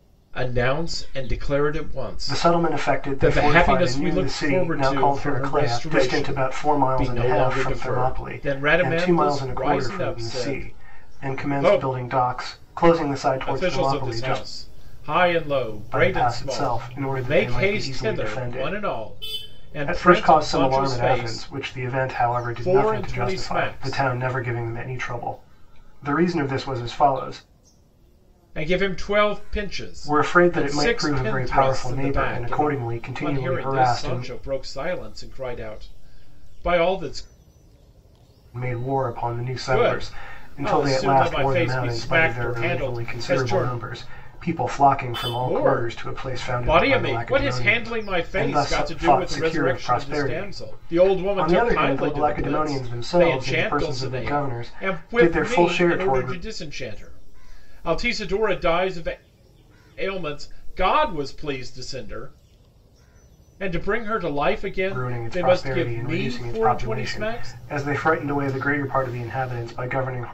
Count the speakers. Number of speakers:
2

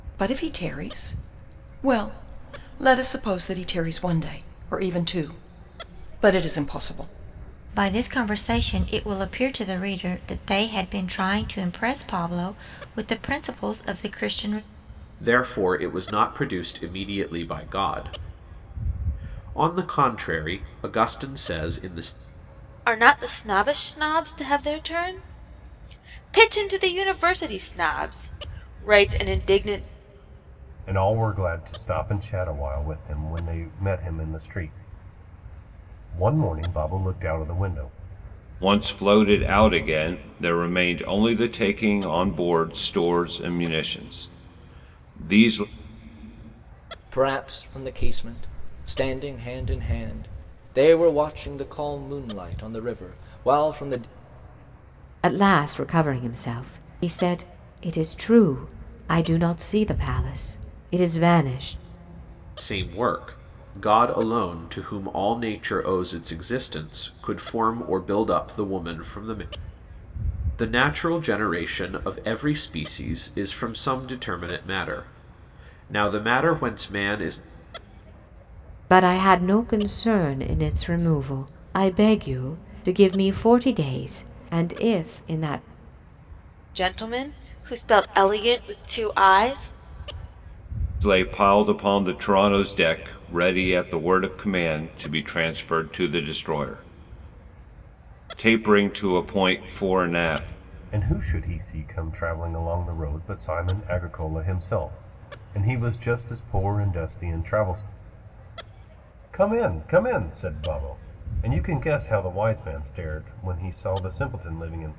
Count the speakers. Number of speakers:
8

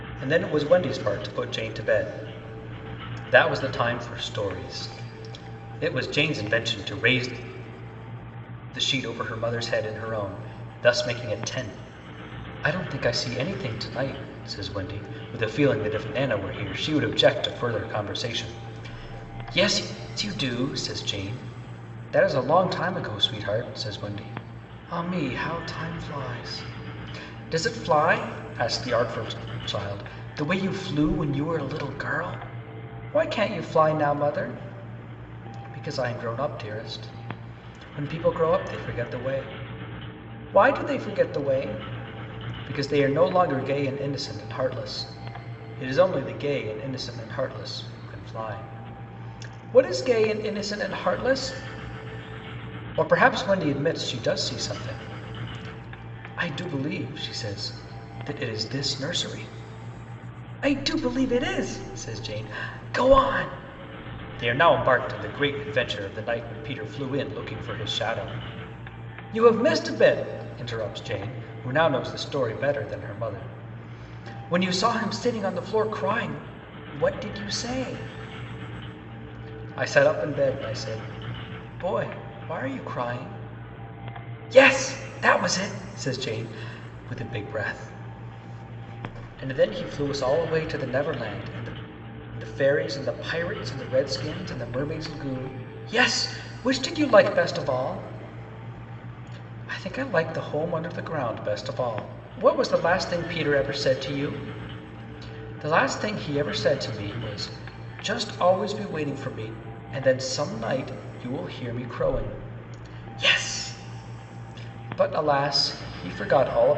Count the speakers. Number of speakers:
1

